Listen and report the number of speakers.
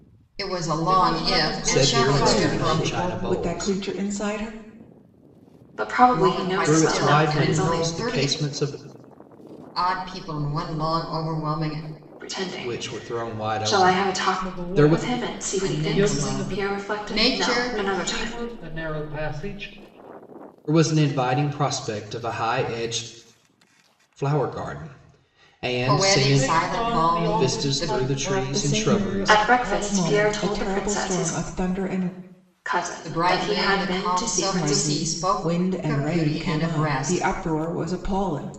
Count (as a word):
five